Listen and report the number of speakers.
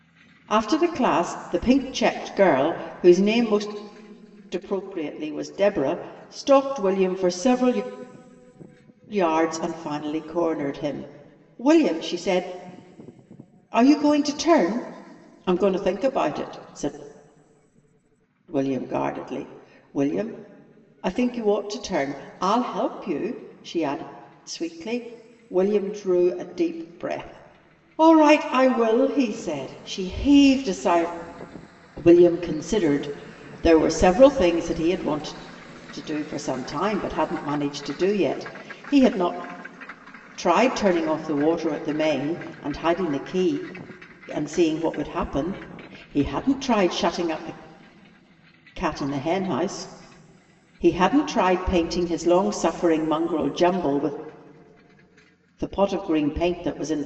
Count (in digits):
1